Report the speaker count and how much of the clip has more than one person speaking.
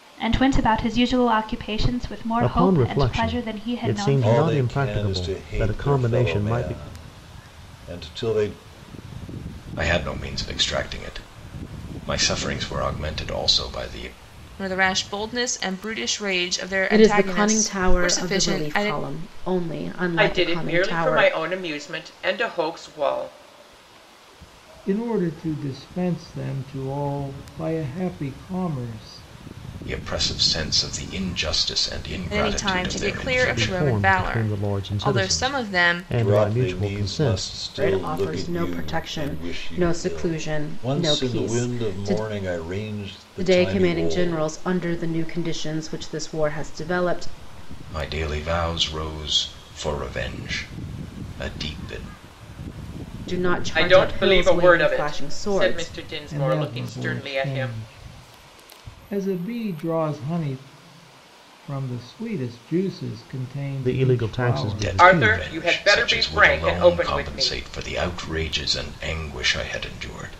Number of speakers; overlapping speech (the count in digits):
8, about 36%